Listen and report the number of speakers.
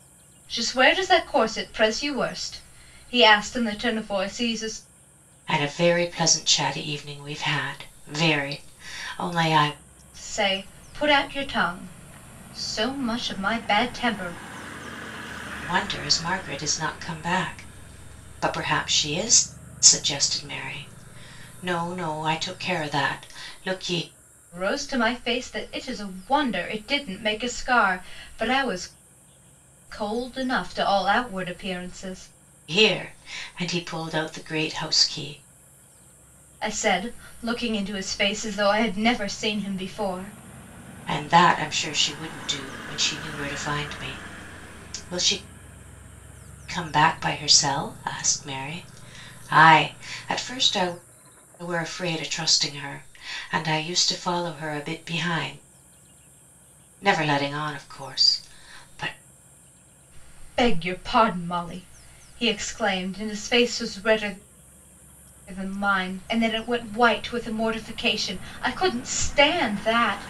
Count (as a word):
two